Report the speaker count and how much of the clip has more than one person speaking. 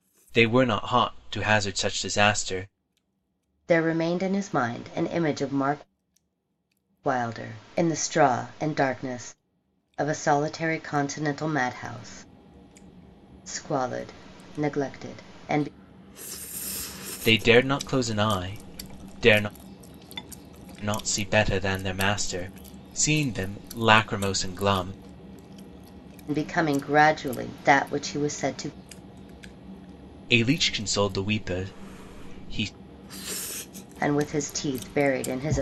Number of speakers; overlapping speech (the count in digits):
2, no overlap